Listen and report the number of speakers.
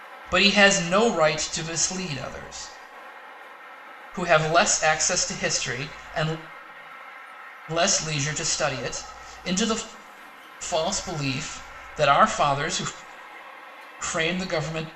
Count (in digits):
1